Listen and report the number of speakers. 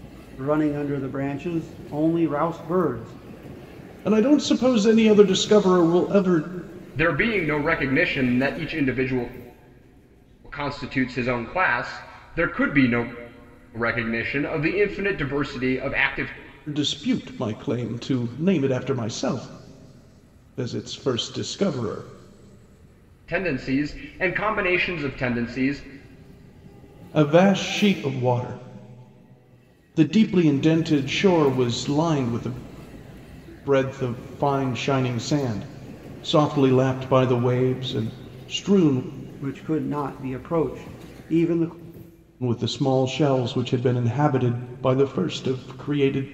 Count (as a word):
three